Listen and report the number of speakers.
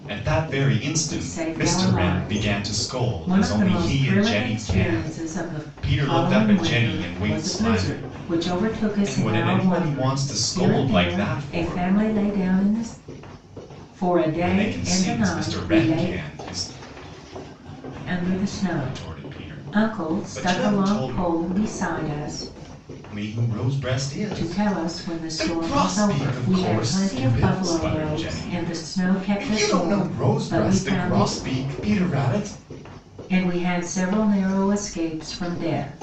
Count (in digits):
2